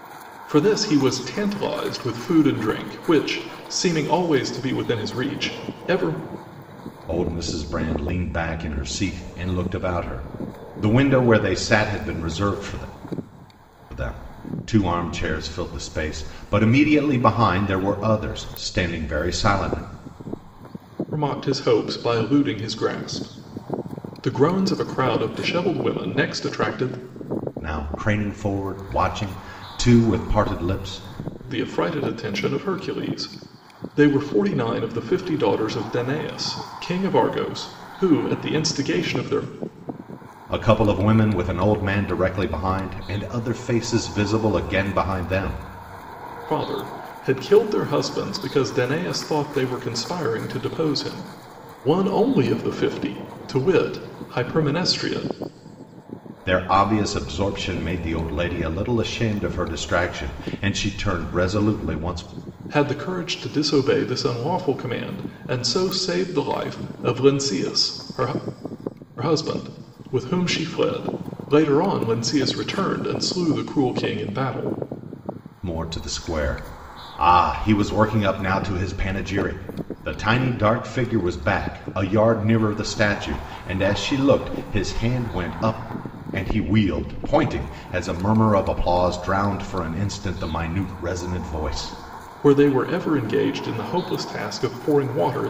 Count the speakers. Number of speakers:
two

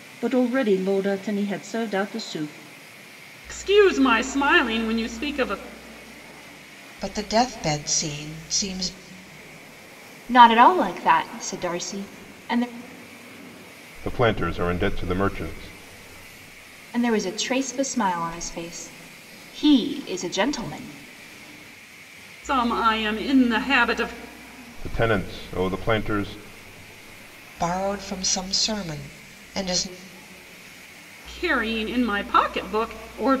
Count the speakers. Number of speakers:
five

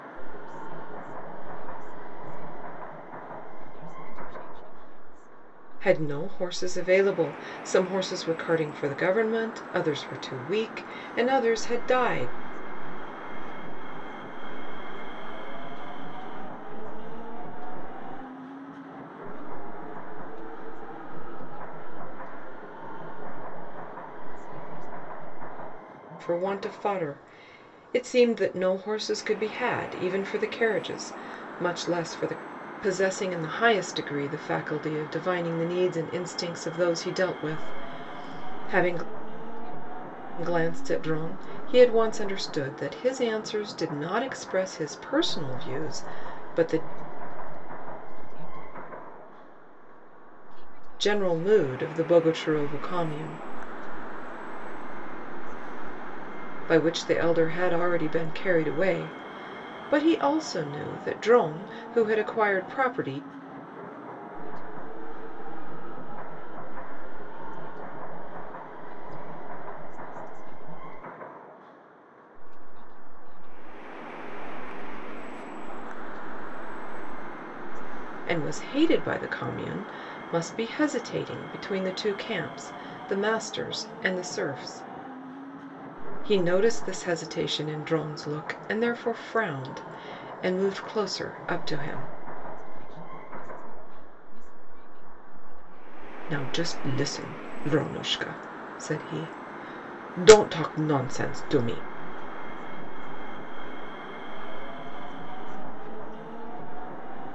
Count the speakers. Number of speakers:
two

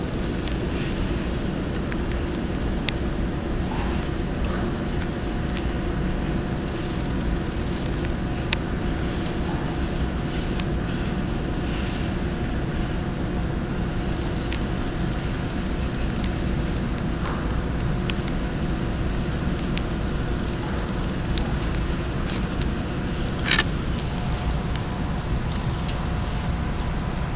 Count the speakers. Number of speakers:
zero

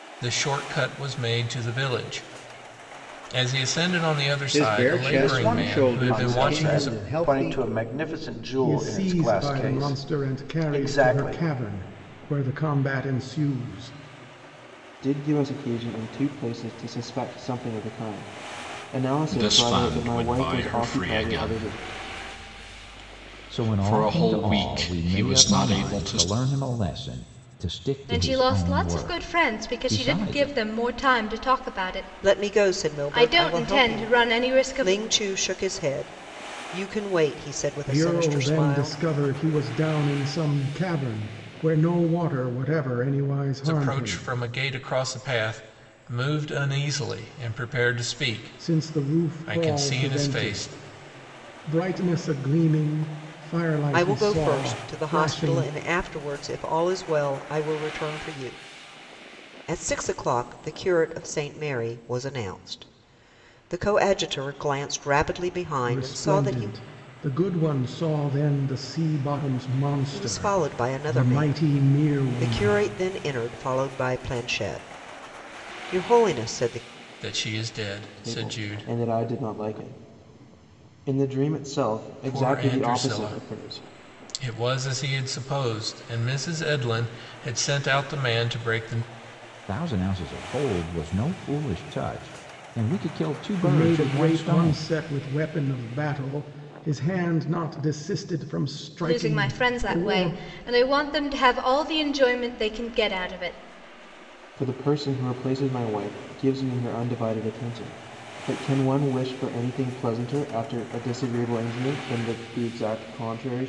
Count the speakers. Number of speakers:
nine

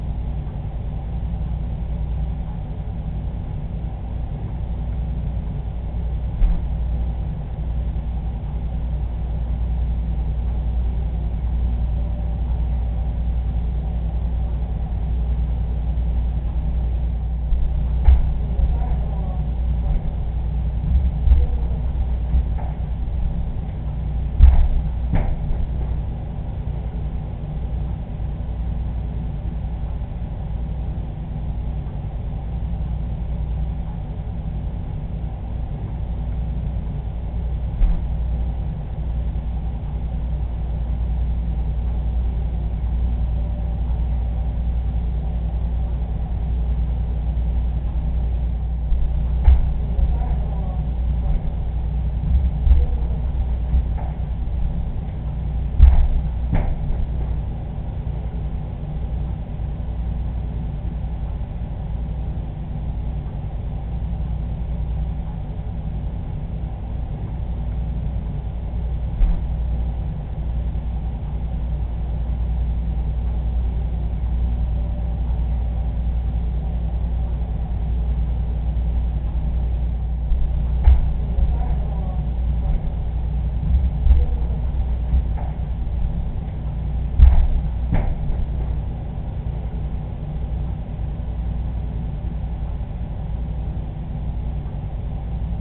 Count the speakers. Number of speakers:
zero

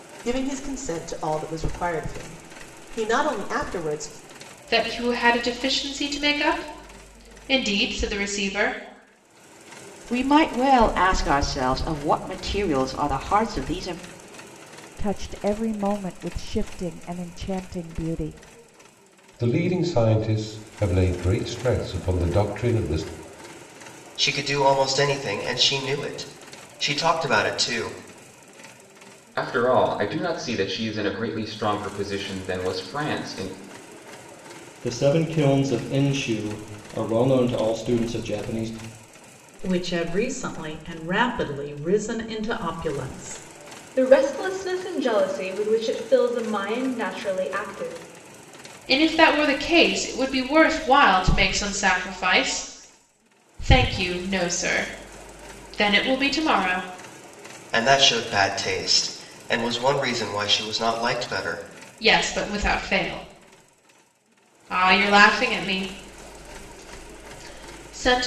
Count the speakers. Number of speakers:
ten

